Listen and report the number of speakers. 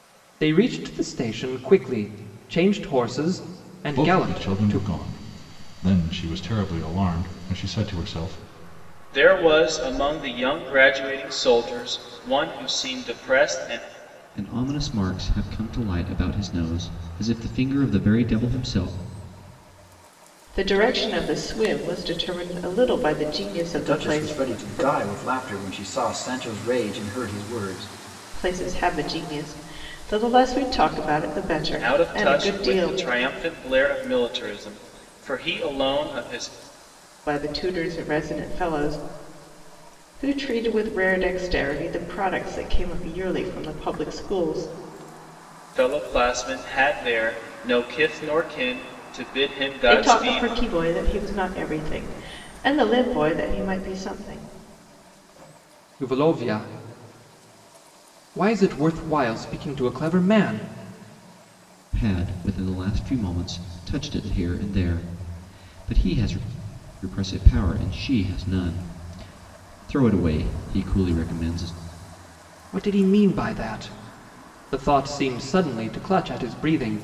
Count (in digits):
6